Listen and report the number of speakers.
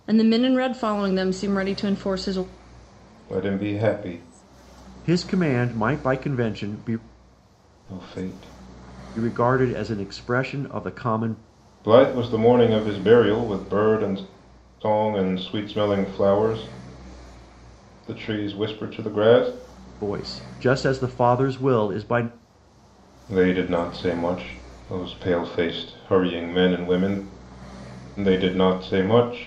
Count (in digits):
3